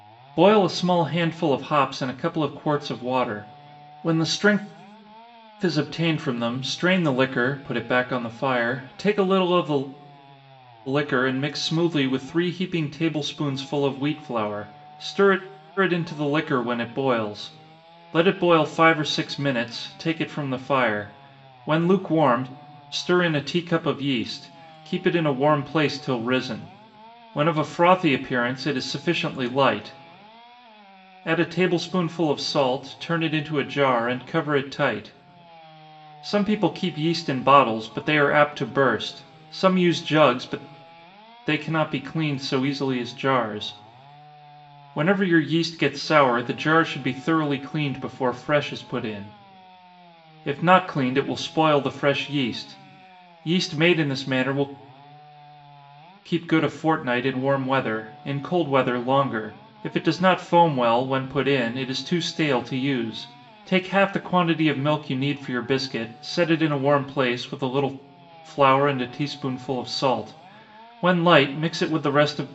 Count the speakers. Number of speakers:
1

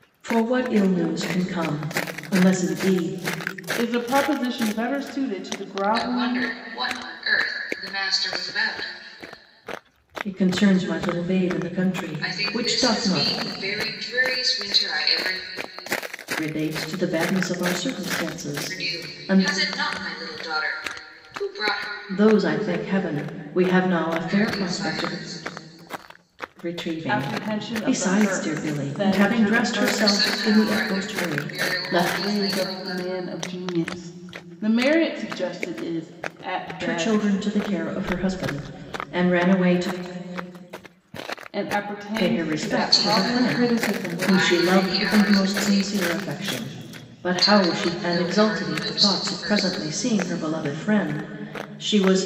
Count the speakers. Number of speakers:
3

